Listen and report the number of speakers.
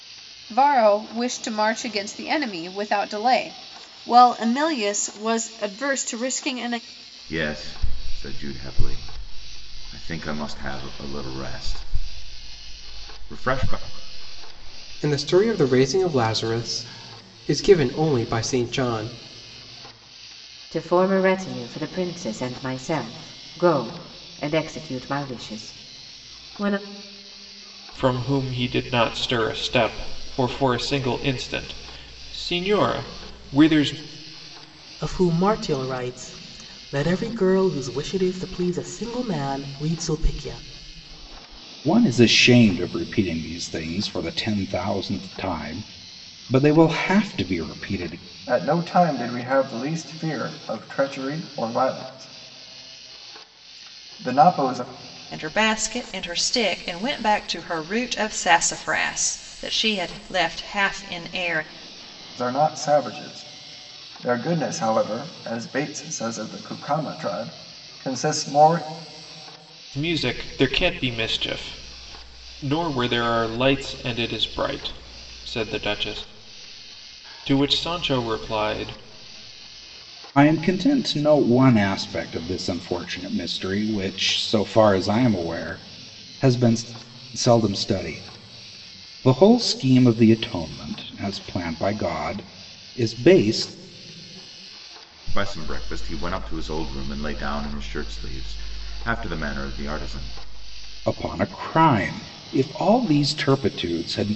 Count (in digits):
9